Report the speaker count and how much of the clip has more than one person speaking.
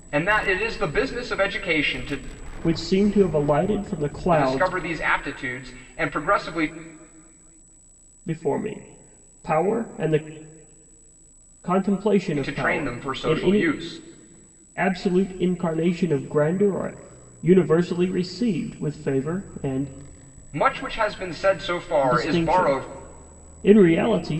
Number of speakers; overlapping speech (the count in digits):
2, about 11%